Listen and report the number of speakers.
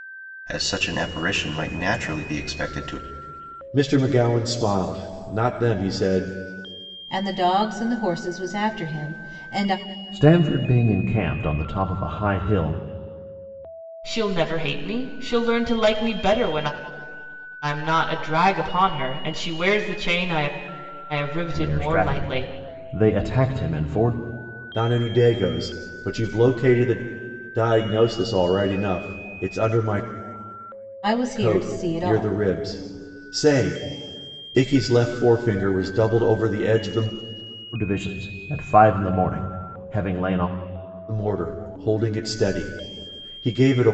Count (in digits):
5